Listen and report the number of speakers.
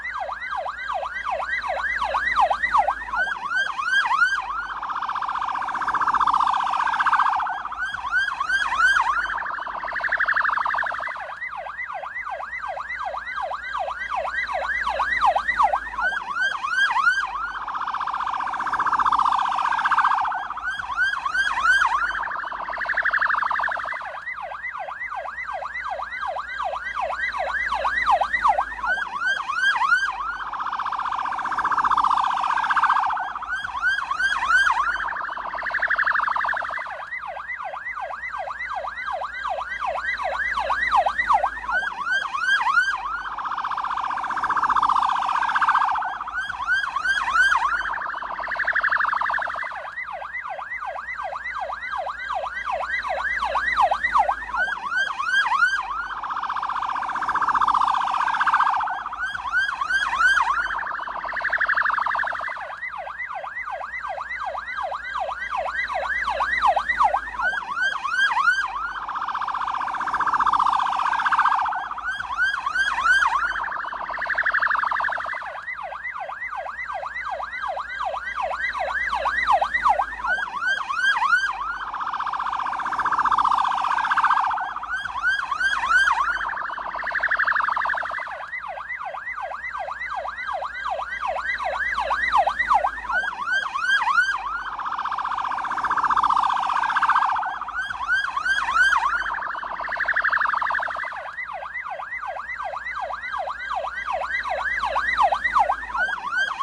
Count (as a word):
zero